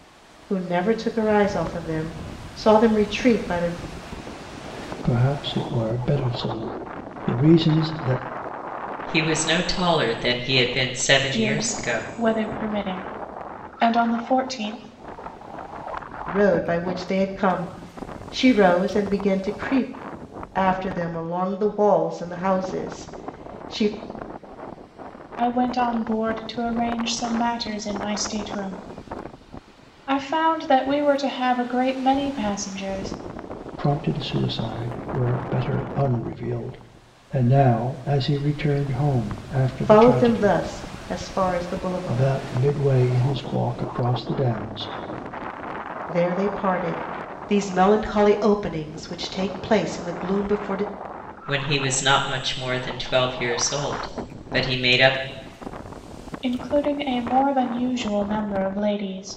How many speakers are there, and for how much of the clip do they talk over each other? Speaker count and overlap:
4, about 3%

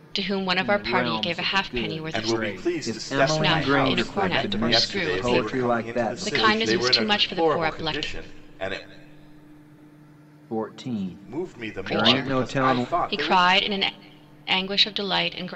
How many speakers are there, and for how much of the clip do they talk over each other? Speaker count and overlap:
3, about 64%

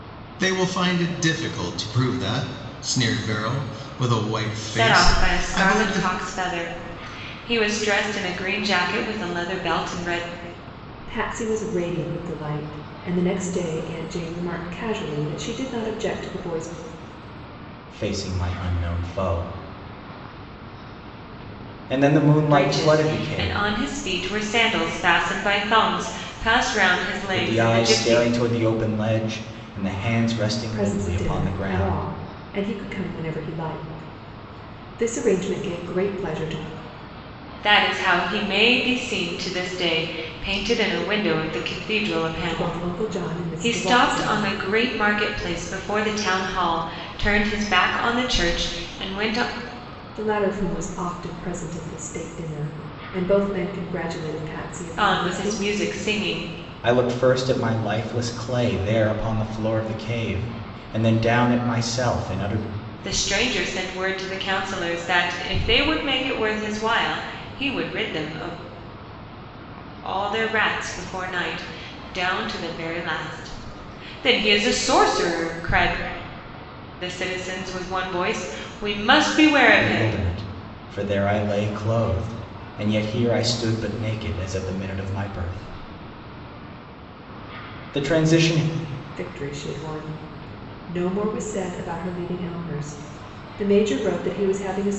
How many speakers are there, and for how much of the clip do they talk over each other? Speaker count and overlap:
4, about 8%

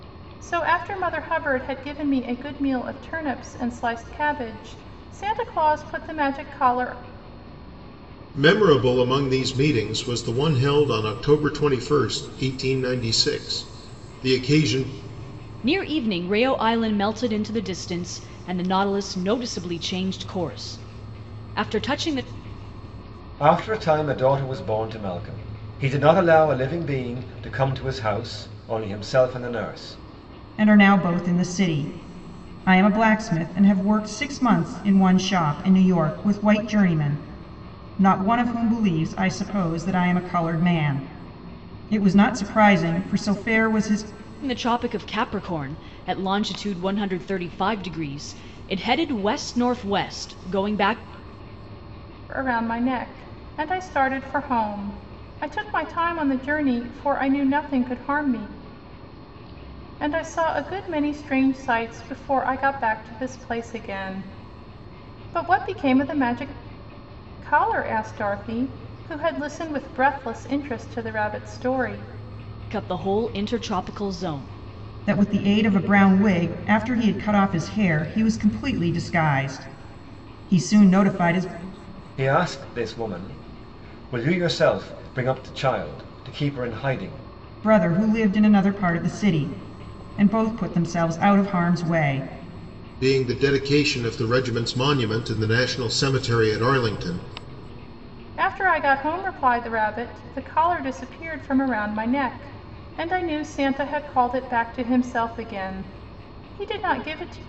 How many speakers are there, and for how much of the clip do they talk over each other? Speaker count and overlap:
5, no overlap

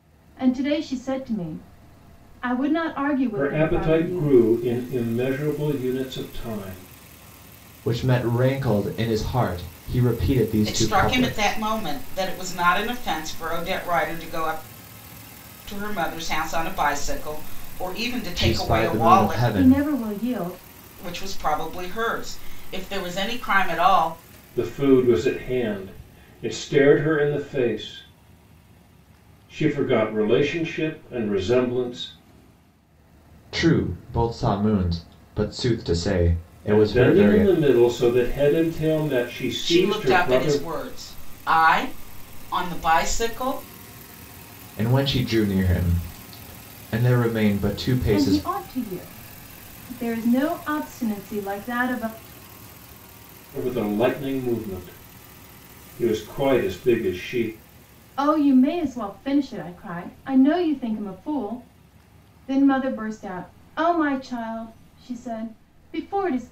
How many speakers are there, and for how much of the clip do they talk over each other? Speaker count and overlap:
4, about 9%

